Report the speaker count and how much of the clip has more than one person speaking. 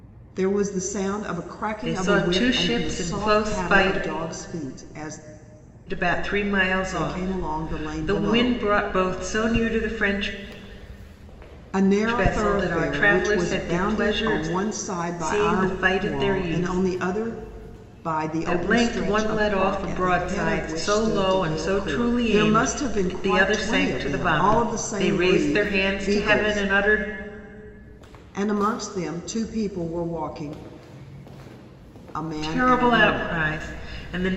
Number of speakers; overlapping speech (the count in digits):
2, about 49%